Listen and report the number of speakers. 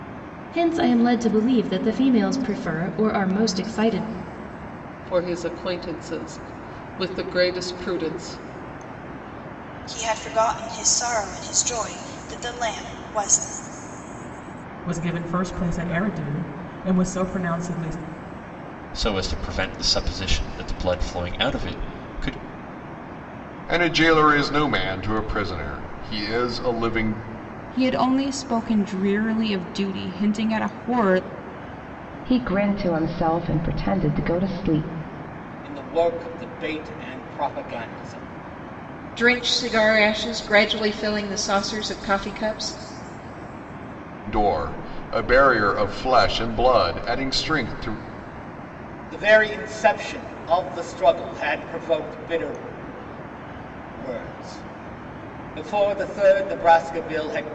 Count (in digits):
10